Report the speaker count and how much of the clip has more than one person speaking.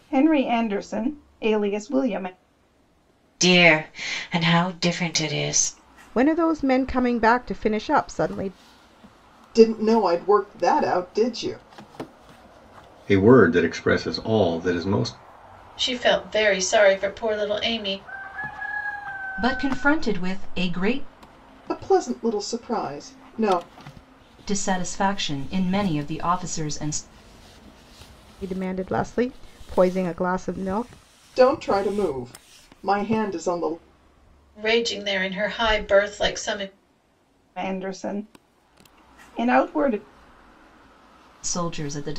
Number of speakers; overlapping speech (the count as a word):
seven, no overlap